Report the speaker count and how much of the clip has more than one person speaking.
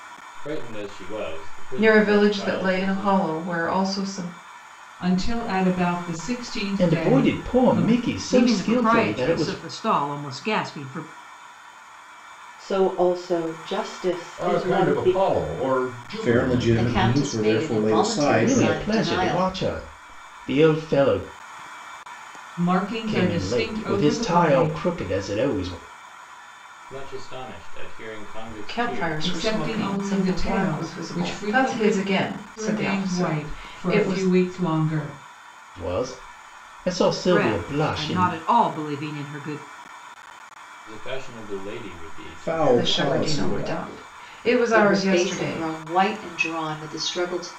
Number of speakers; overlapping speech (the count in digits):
9, about 39%